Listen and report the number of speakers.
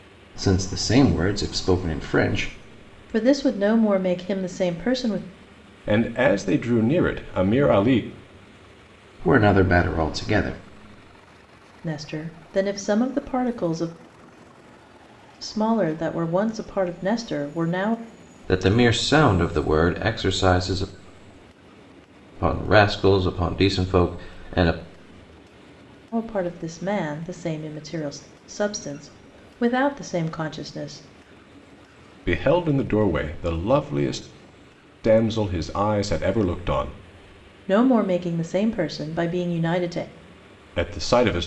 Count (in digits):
3